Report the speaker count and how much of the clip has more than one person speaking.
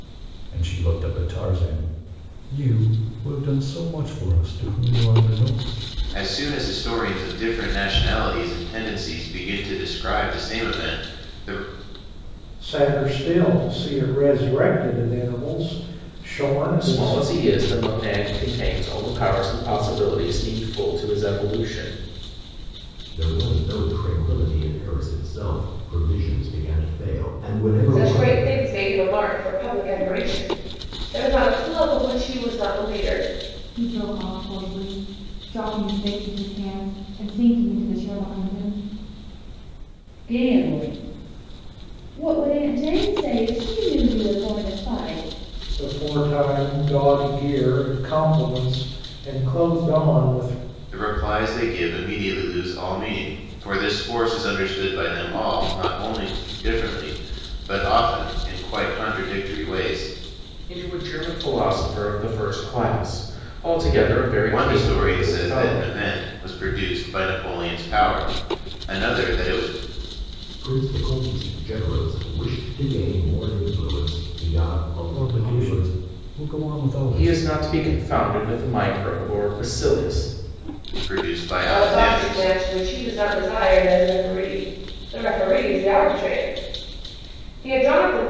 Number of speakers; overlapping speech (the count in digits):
8, about 5%